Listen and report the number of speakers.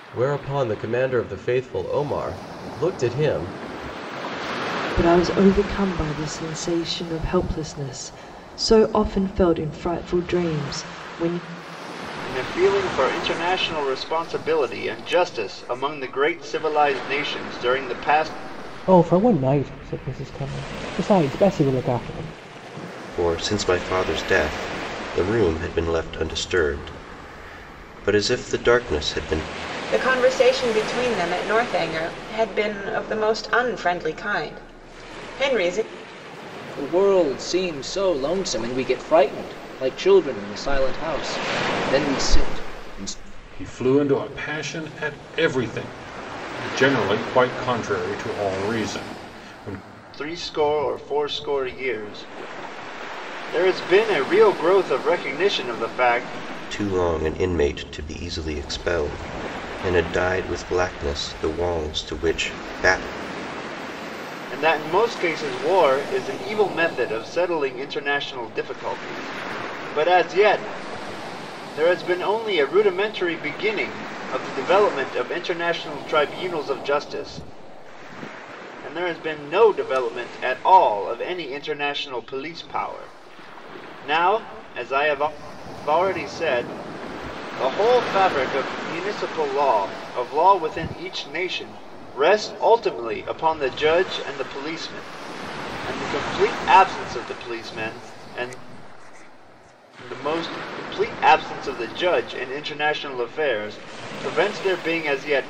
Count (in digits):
8